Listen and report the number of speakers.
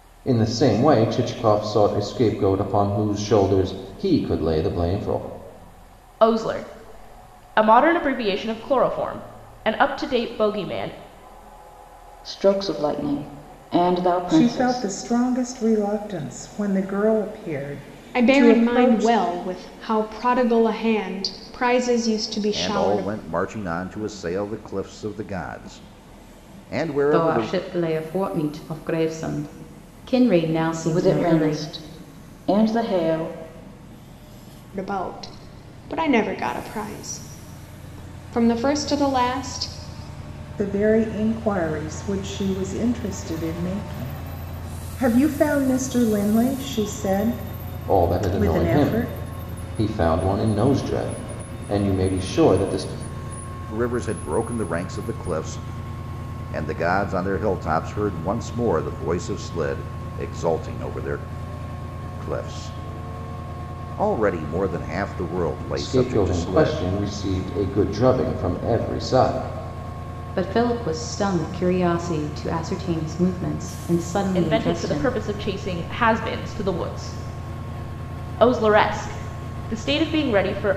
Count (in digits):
7